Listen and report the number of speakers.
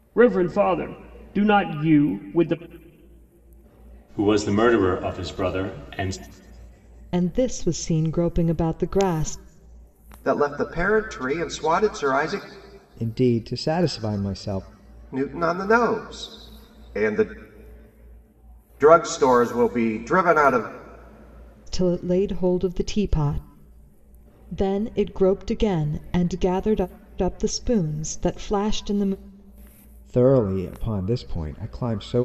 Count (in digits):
5